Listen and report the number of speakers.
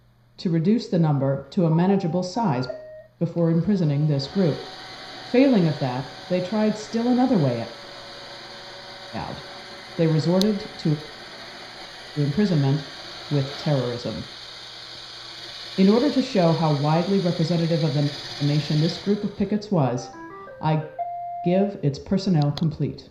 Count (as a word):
one